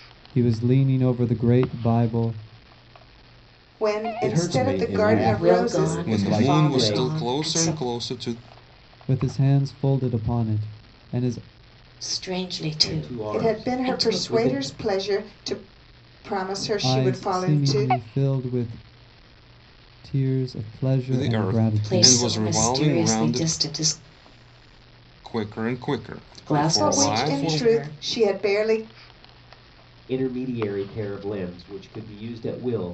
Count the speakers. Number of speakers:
6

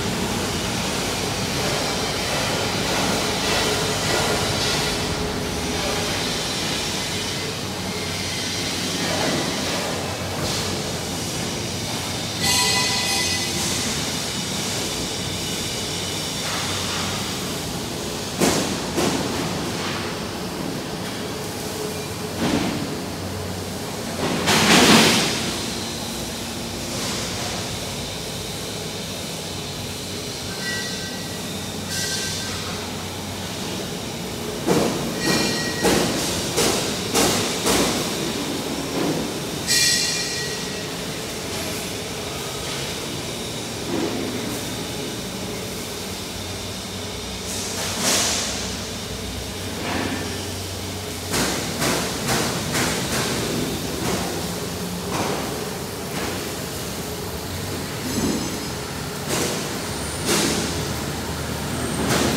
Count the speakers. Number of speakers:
0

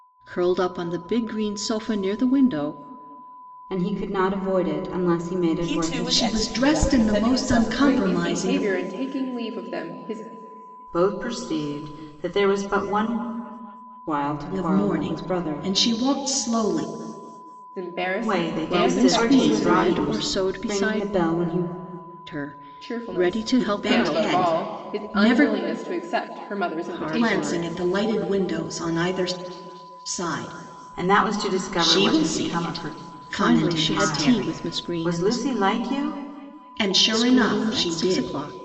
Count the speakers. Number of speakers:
6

